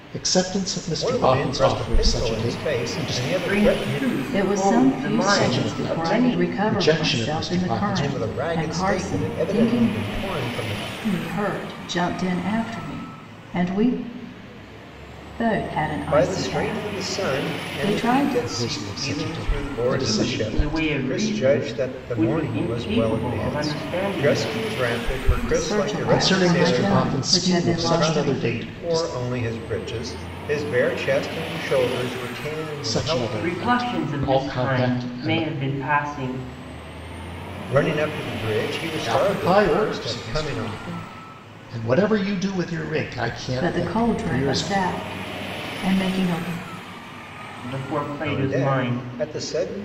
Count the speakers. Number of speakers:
4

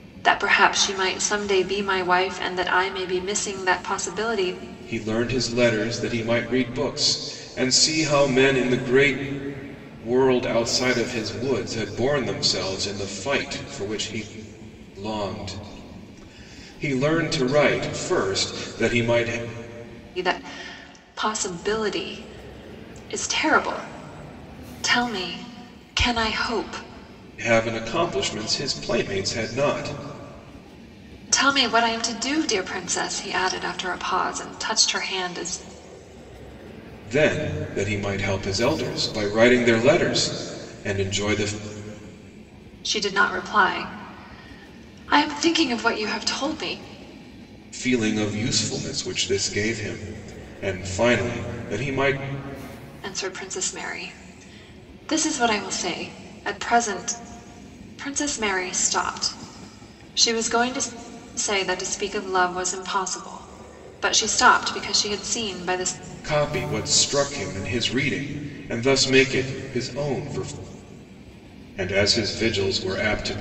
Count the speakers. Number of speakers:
2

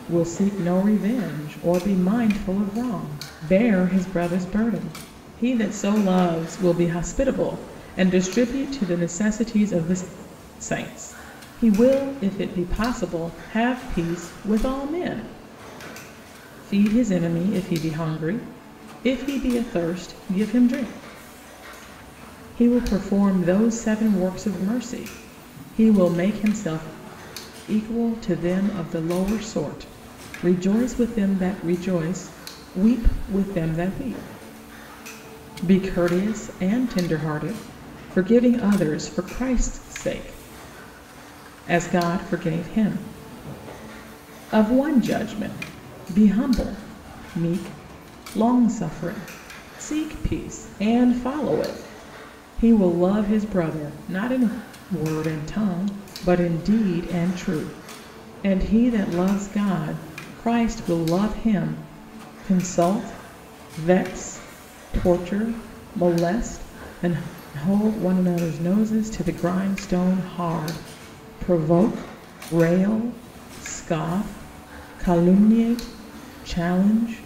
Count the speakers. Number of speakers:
1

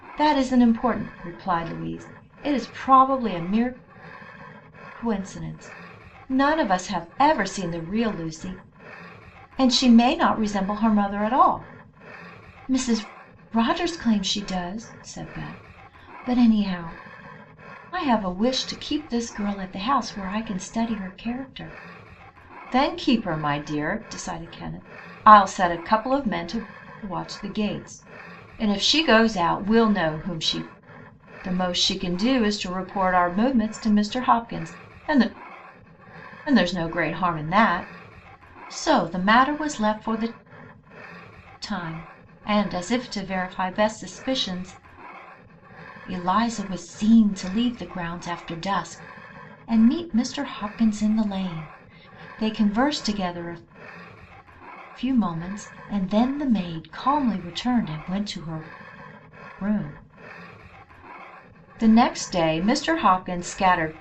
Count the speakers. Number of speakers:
1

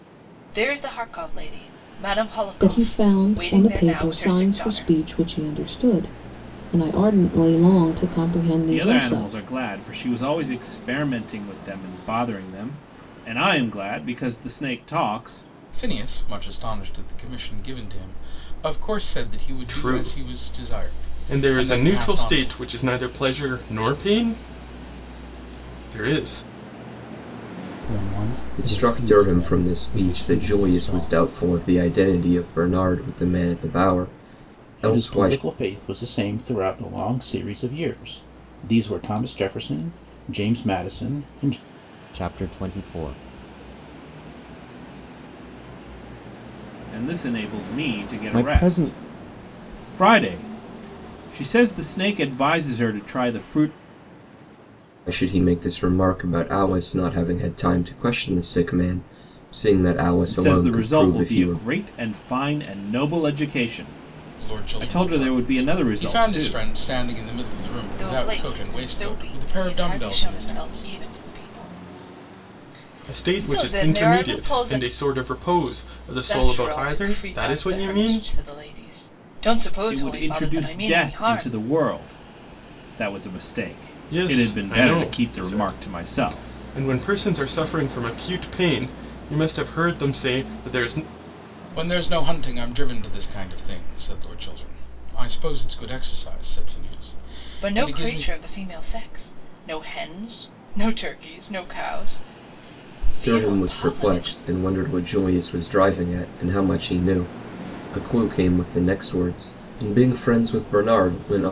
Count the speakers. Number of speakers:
9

